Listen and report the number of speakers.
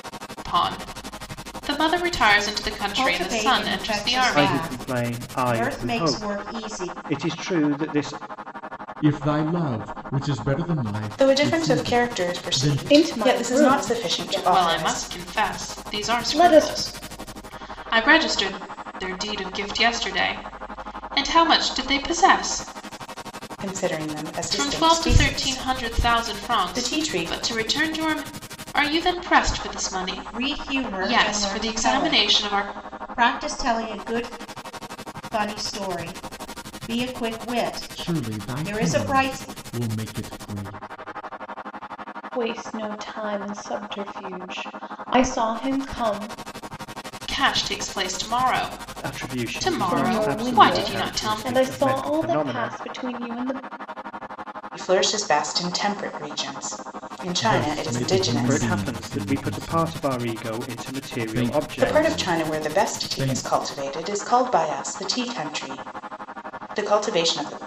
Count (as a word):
six